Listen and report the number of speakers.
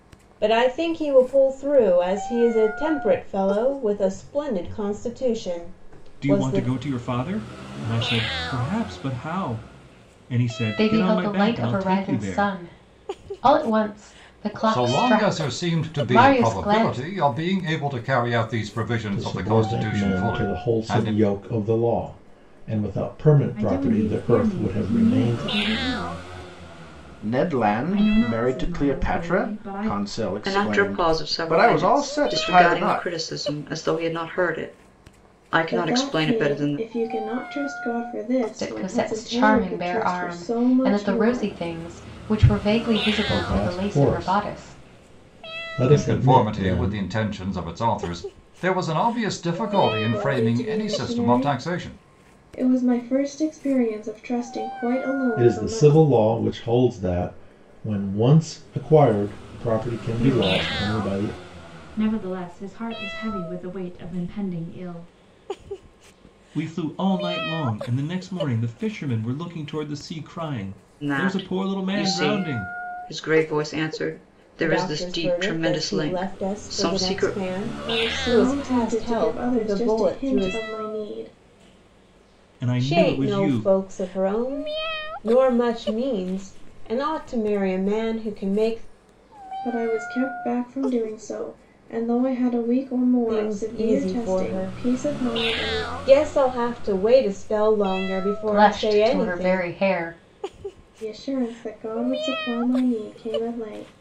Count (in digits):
9